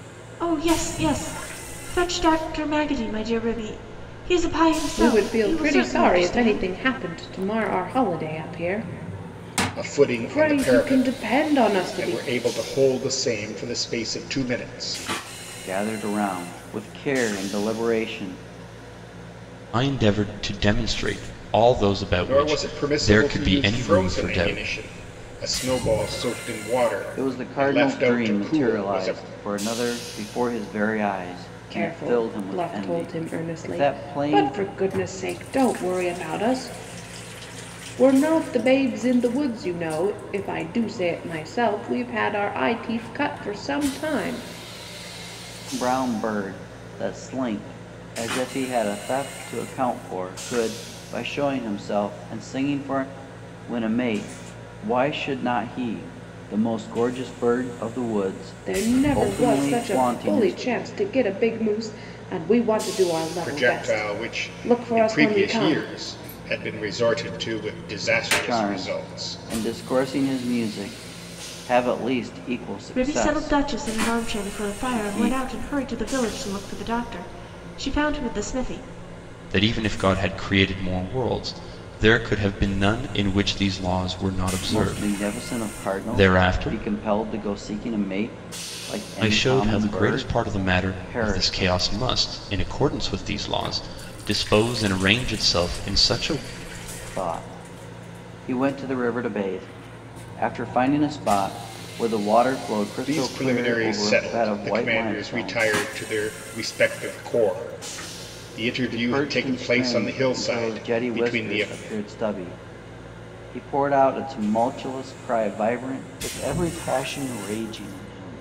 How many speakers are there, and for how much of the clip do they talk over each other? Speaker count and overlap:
five, about 25%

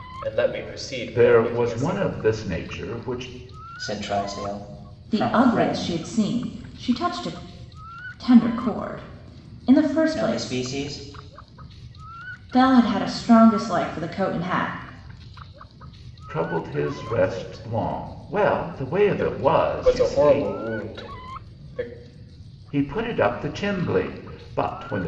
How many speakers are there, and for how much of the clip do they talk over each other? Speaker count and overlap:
four, about 23%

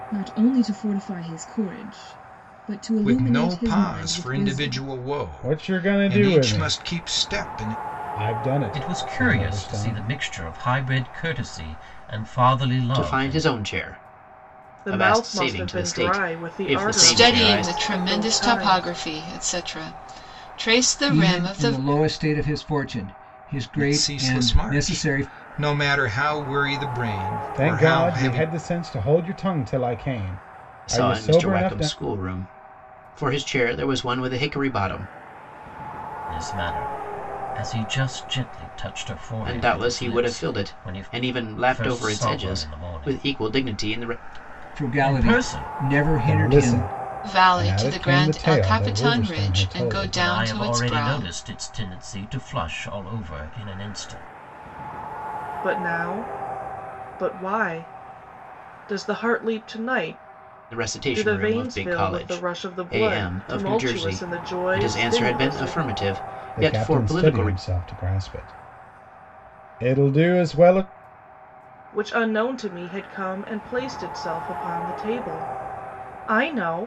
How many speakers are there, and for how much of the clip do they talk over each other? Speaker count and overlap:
eight, about 39%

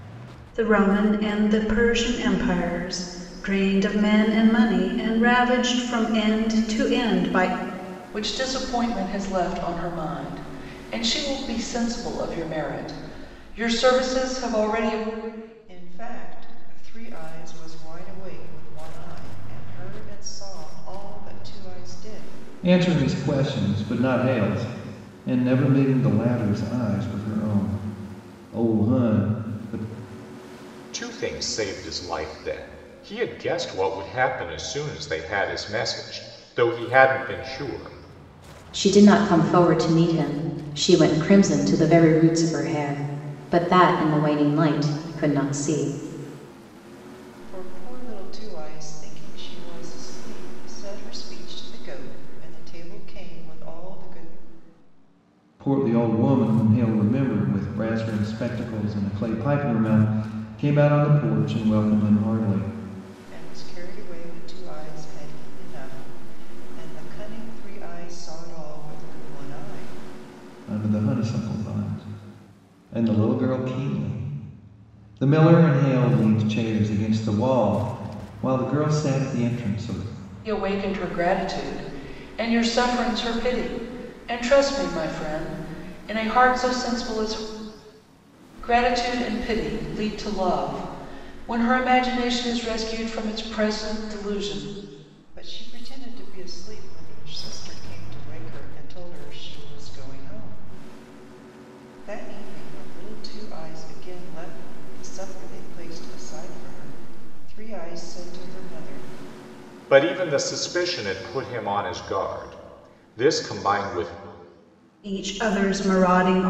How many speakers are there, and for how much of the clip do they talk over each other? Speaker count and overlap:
six, no overlap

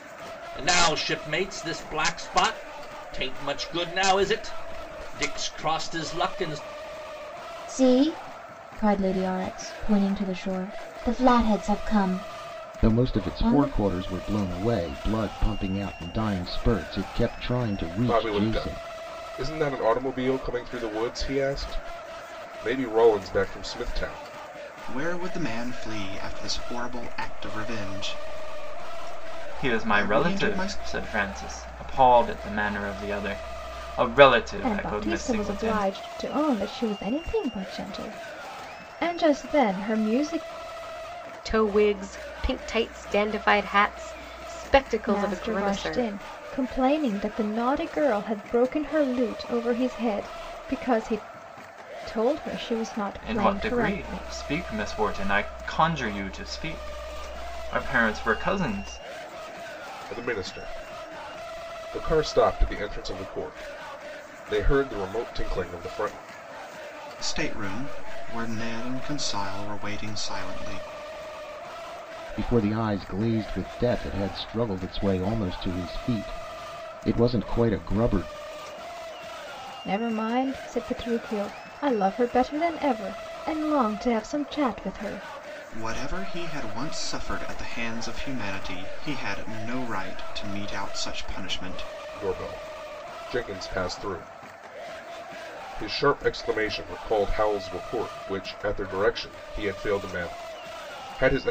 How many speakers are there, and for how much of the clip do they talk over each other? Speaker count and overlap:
eight, about 6%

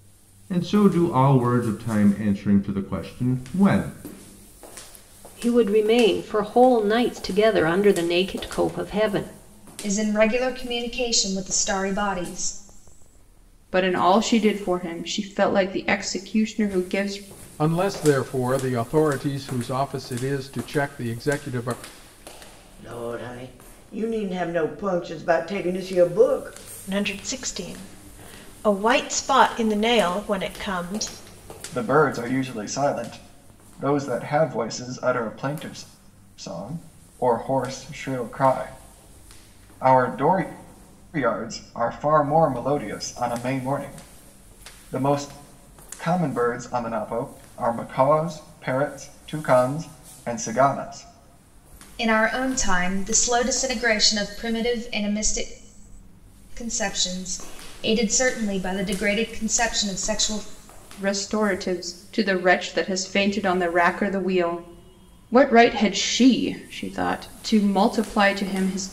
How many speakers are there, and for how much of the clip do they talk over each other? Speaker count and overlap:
eight, no overlap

